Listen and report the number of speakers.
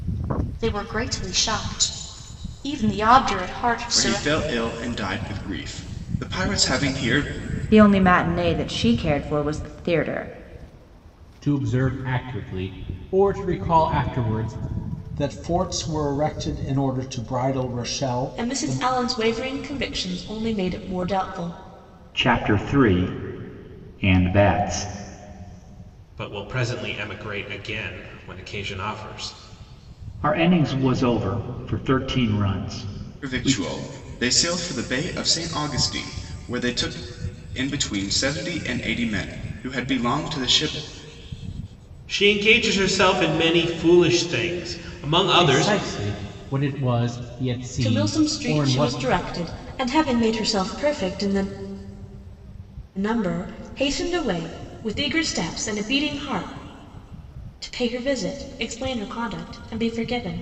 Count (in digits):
8